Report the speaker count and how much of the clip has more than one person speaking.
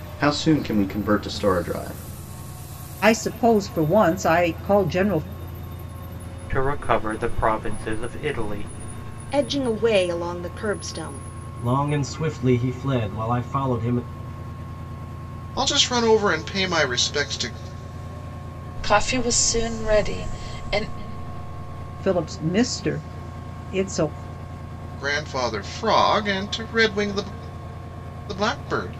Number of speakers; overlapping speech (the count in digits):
7, no overlap